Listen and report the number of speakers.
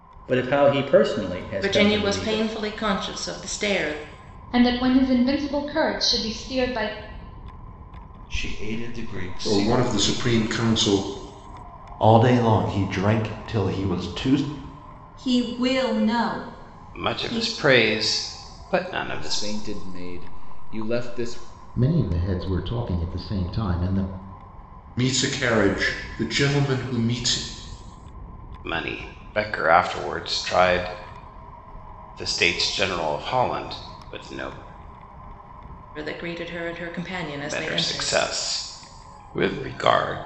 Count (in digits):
10